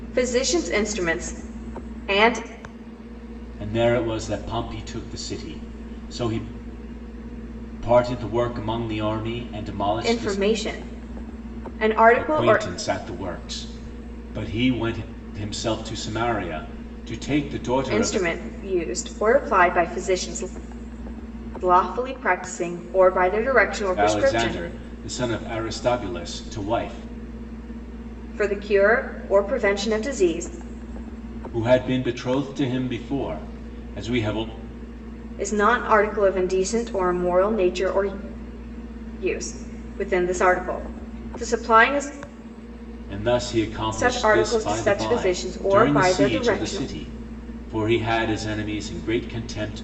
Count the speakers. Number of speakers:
two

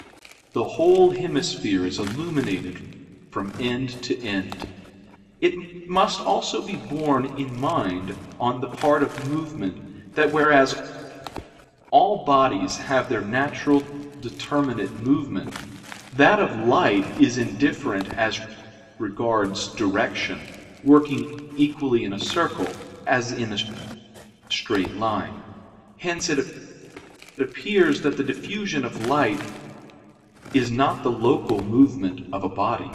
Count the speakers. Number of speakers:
one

